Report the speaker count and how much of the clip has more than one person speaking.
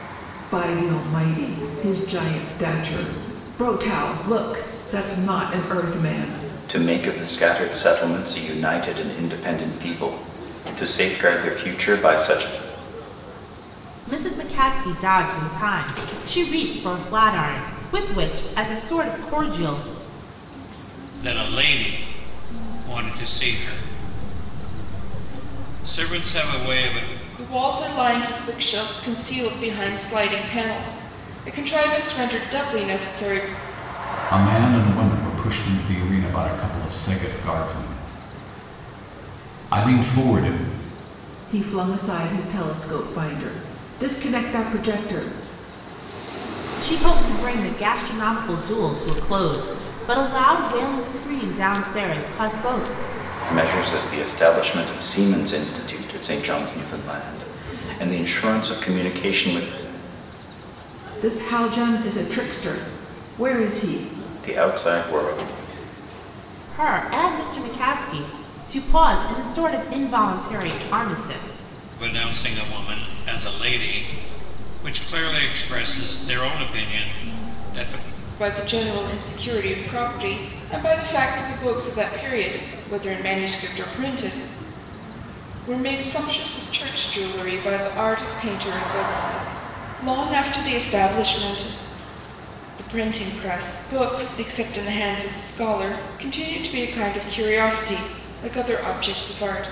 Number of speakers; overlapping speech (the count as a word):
six, no overlap